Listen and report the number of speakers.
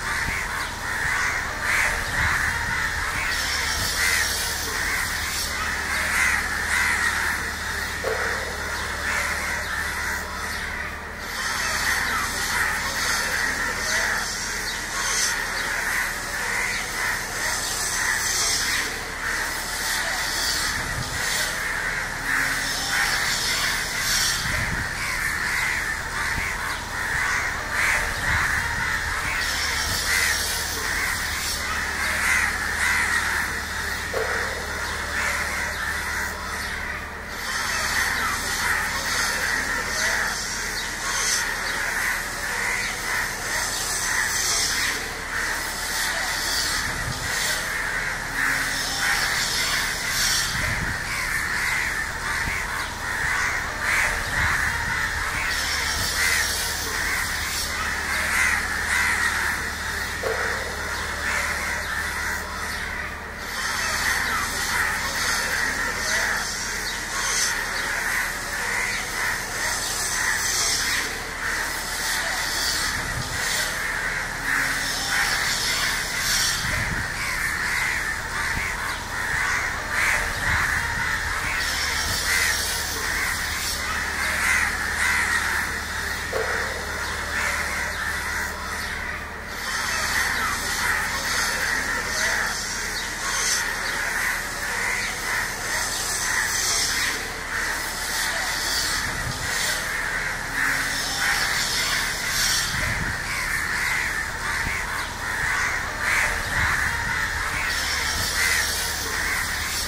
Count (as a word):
zero